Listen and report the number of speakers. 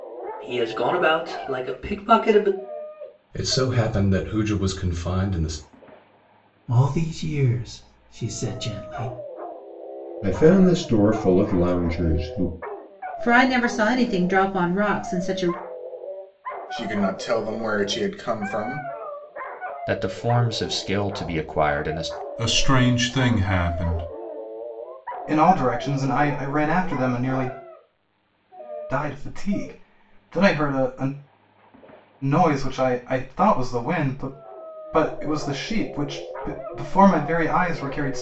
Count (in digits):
9